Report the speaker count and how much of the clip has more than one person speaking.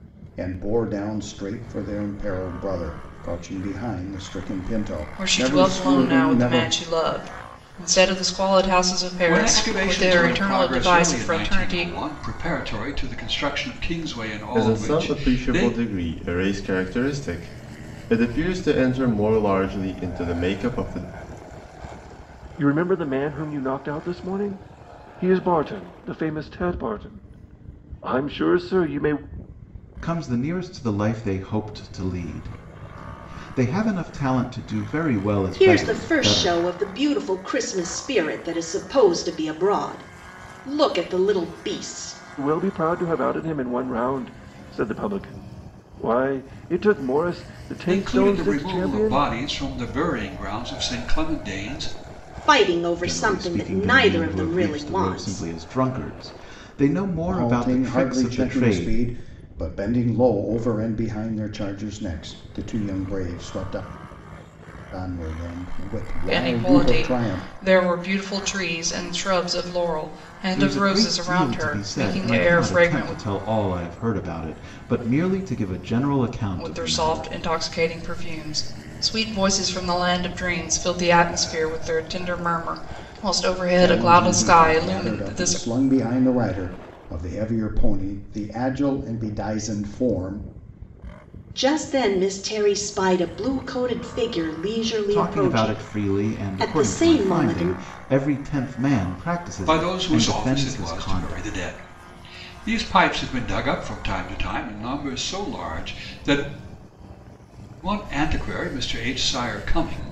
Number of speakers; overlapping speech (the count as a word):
seven, about 21%